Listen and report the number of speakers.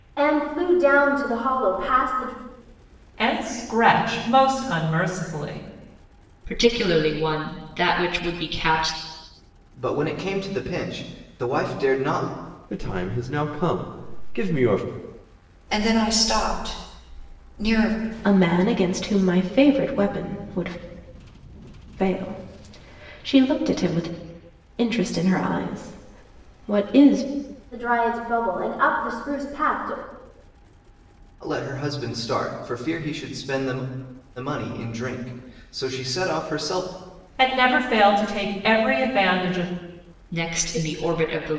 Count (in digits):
7